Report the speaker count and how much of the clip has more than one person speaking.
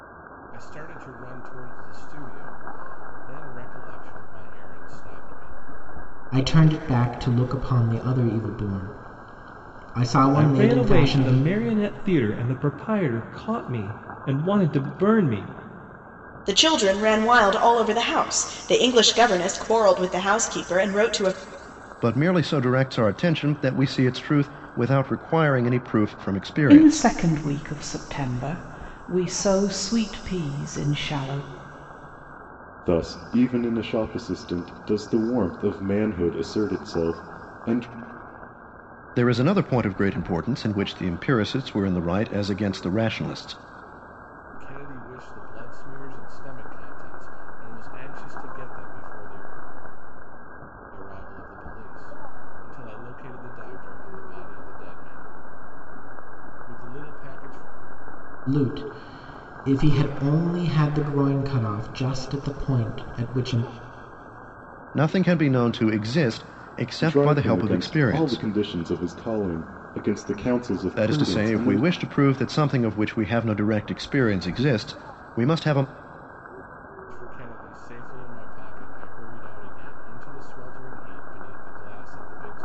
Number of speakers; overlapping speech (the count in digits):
7, about 5%